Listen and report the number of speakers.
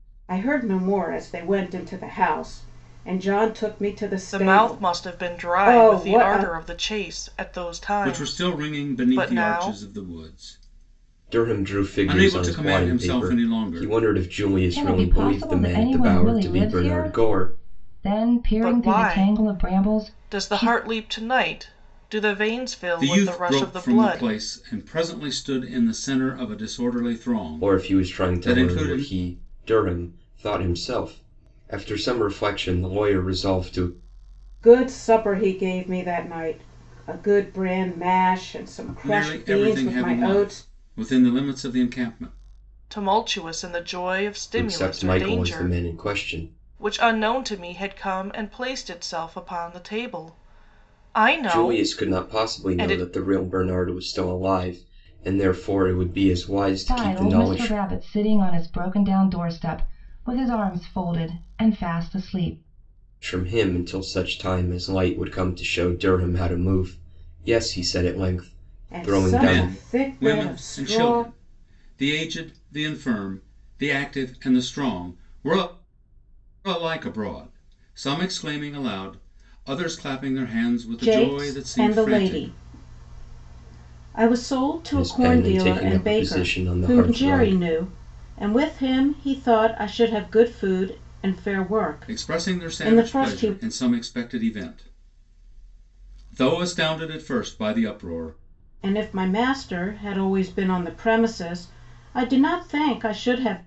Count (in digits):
5